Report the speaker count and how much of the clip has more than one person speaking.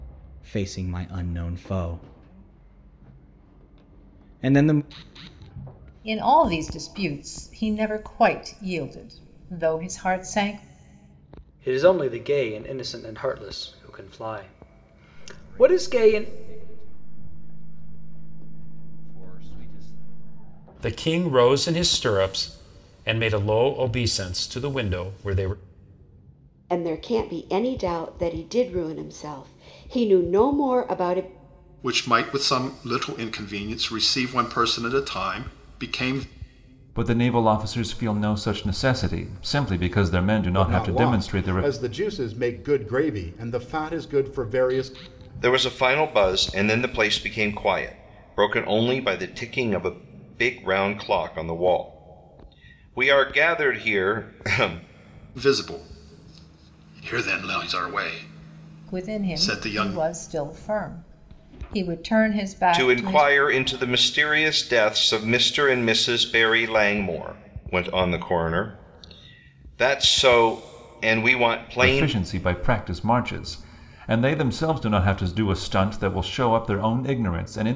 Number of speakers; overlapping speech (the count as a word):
ten, about 6%